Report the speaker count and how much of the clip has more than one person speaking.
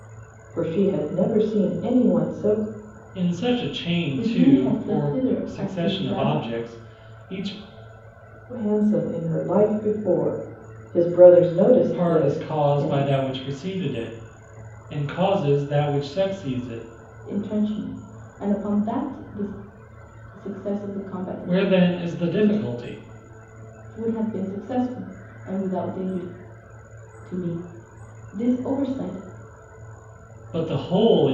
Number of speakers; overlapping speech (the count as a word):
three, about 14%